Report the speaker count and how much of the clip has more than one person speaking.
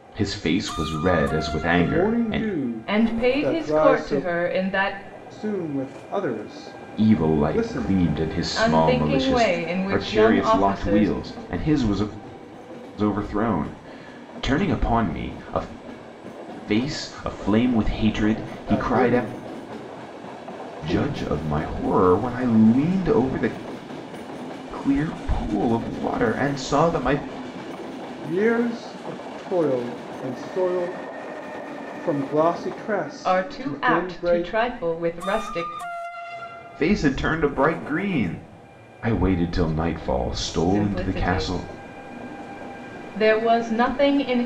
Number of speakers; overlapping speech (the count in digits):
3, about 20%